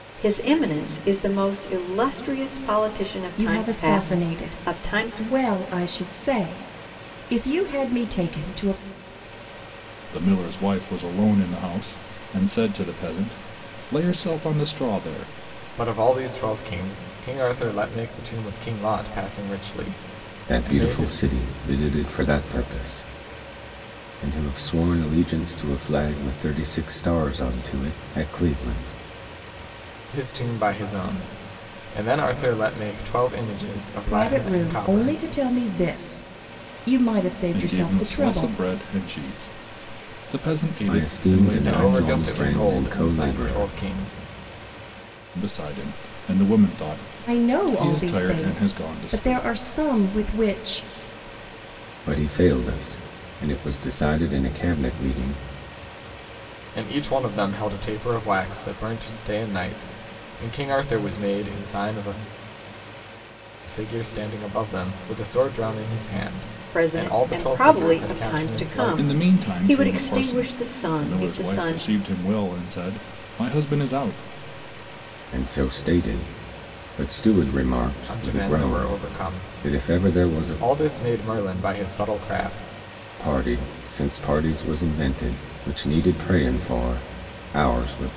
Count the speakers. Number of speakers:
five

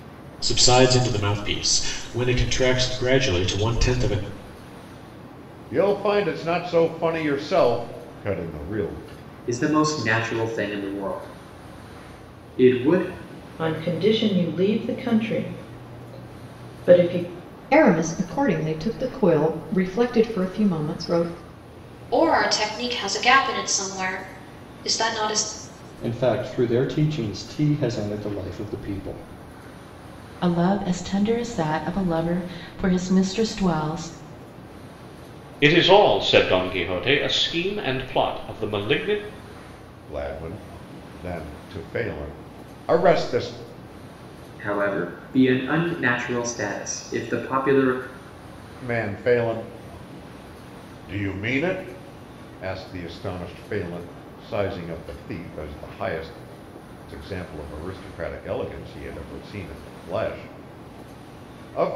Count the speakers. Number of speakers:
nine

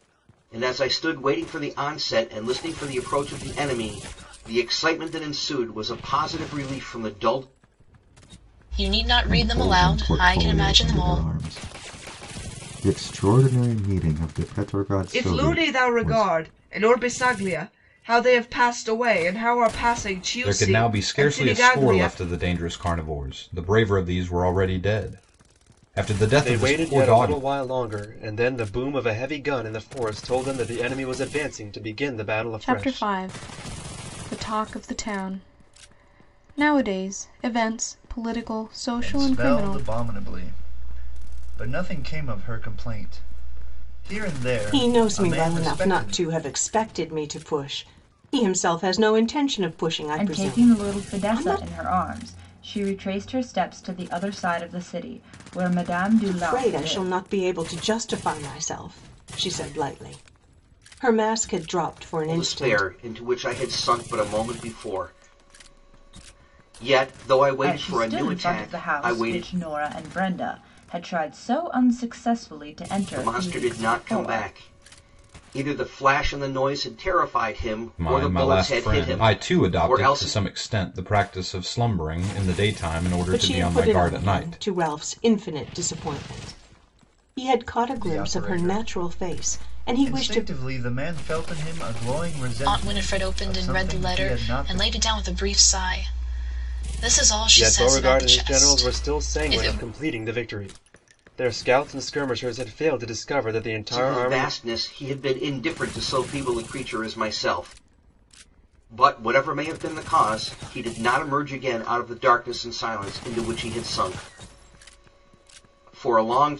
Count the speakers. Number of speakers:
ten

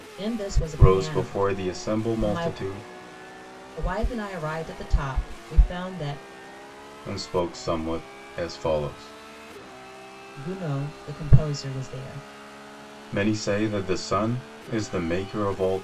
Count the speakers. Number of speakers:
two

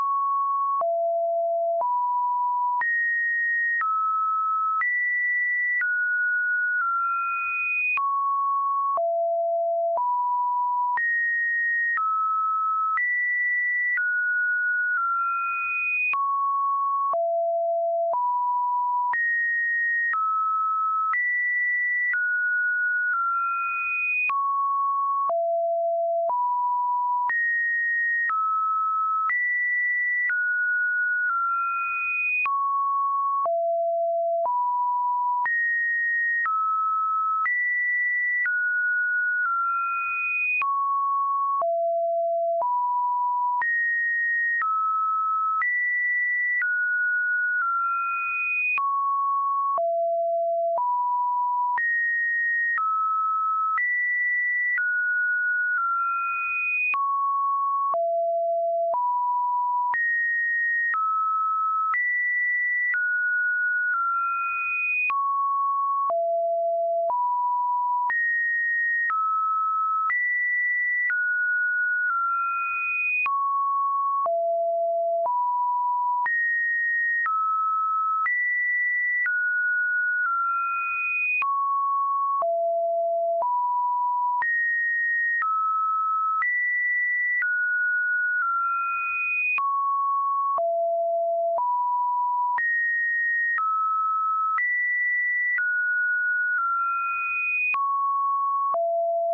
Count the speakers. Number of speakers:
zero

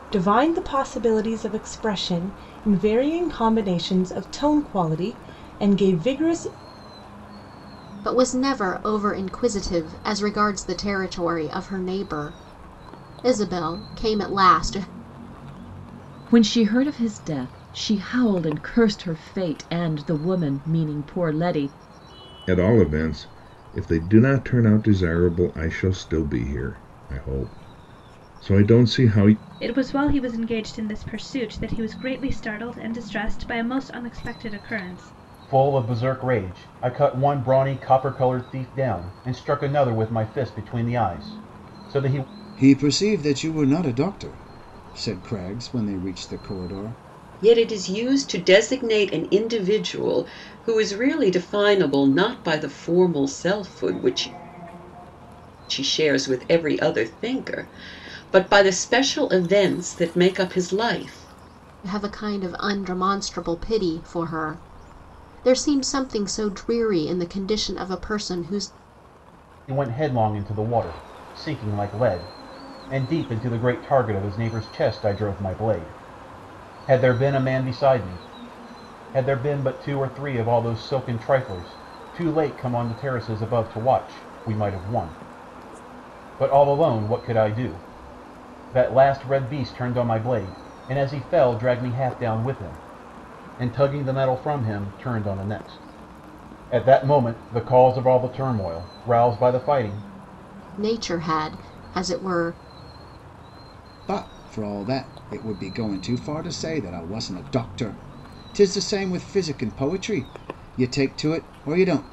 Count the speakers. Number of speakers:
eight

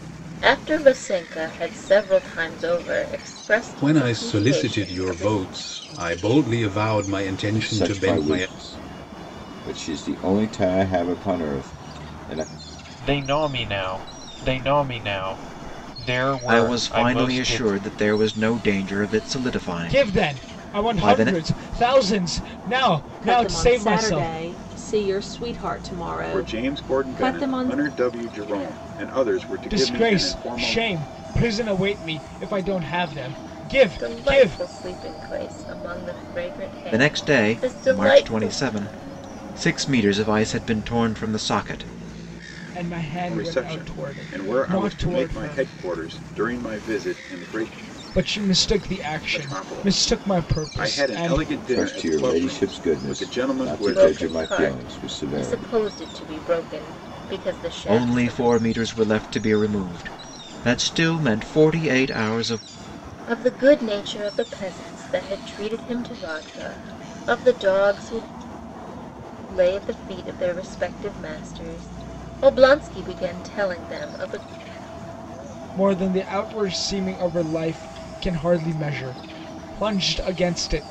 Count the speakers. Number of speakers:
eight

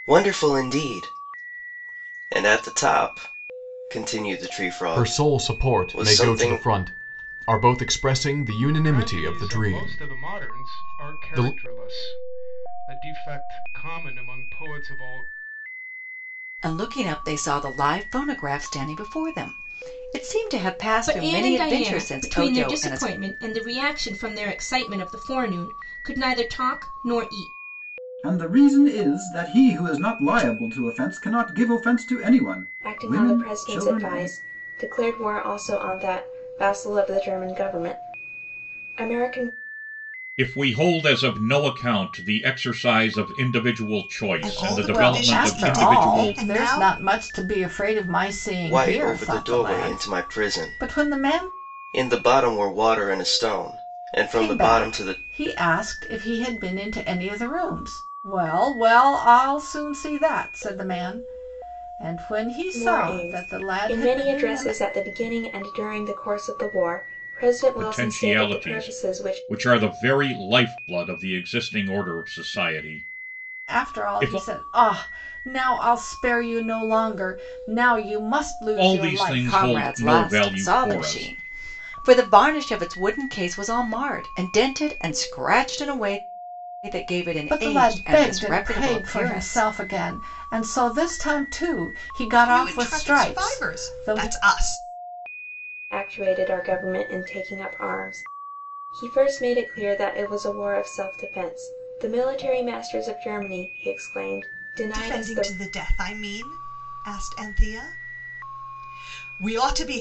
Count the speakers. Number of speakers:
ten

